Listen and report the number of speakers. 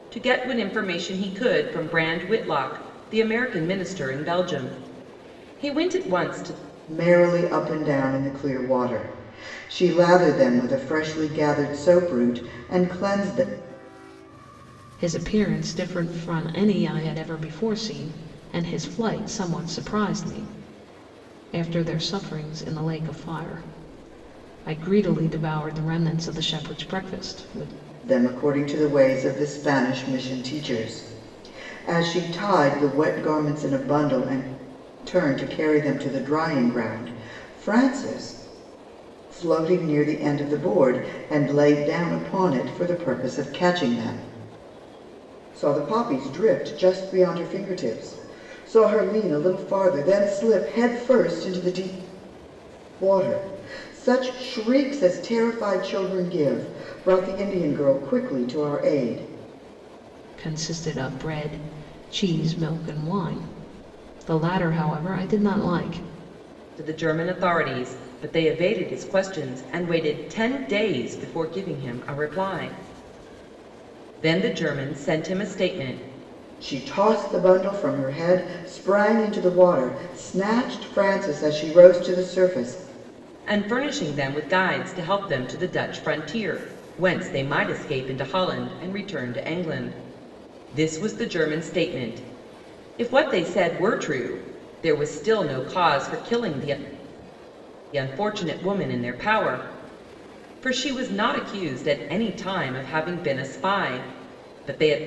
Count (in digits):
3